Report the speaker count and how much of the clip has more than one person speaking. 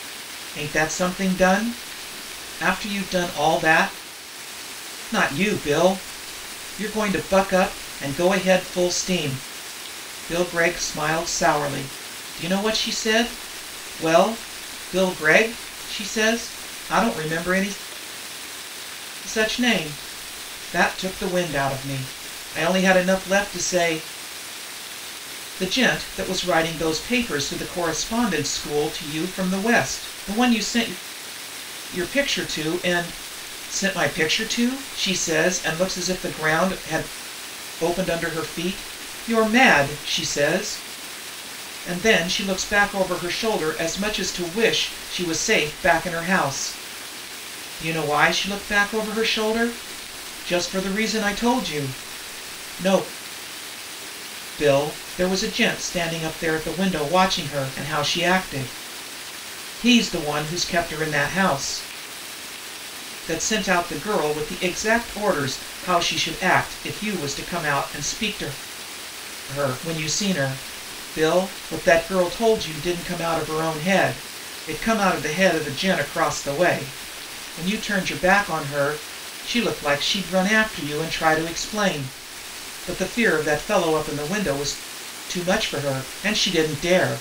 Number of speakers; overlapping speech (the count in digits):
1, no overlap